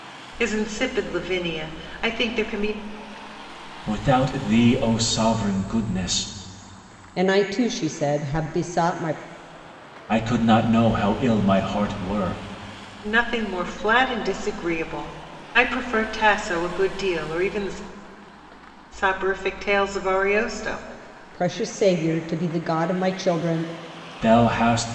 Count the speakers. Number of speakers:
3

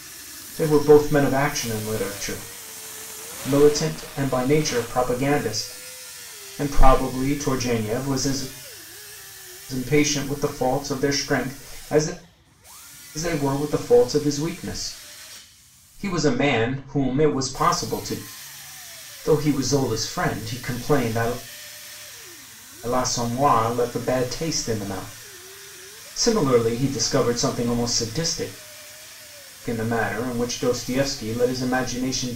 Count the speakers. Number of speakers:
1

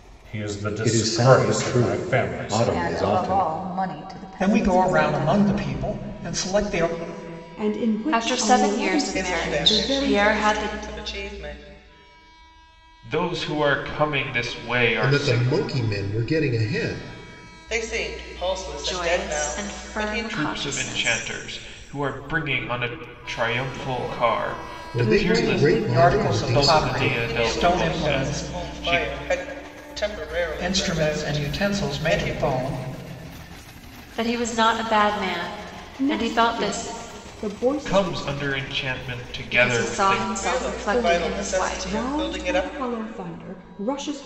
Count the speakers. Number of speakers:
9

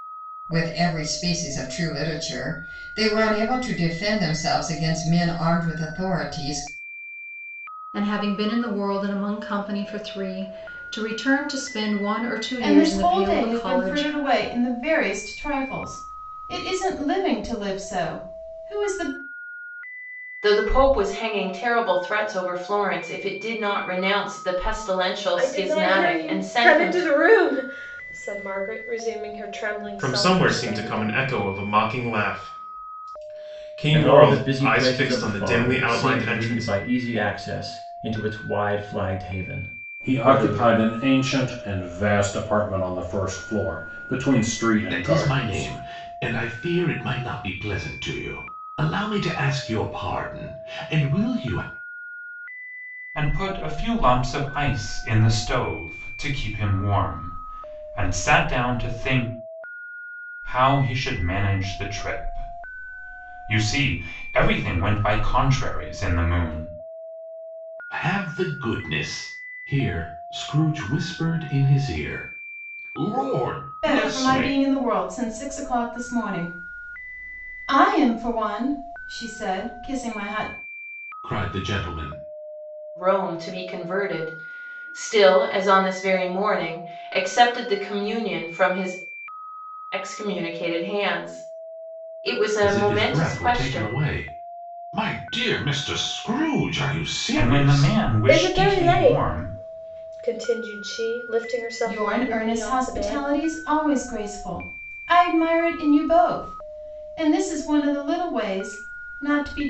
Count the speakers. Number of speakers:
10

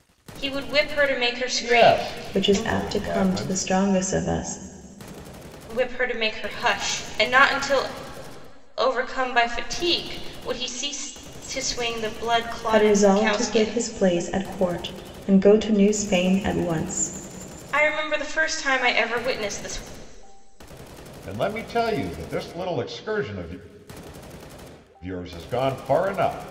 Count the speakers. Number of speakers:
3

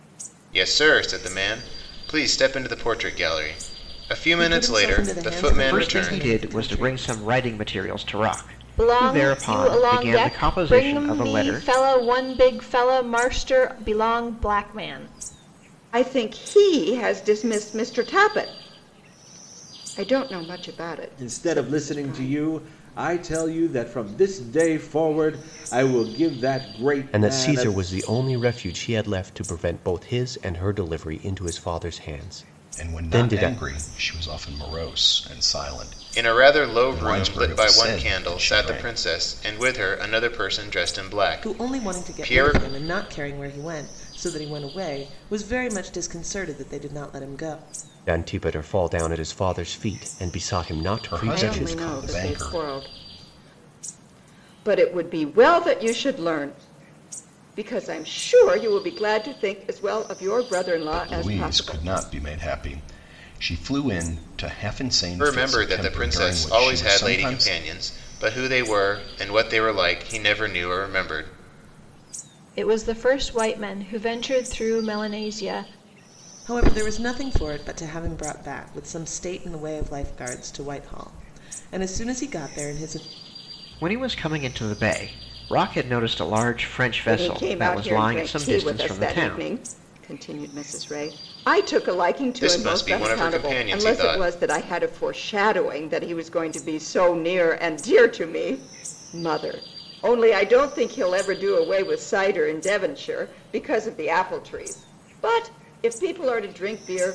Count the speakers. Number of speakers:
8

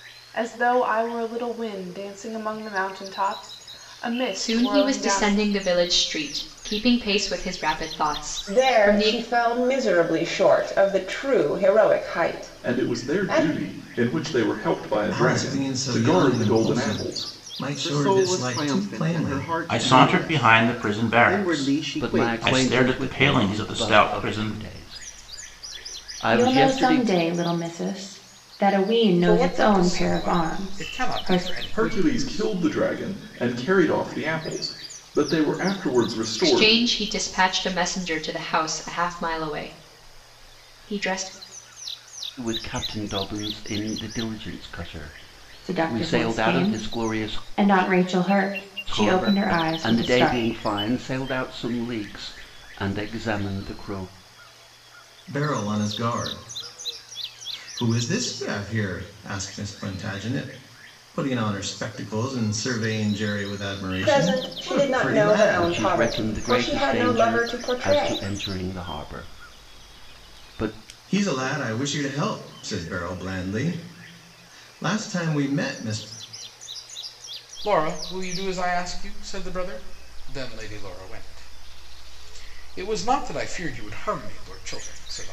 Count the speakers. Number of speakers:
10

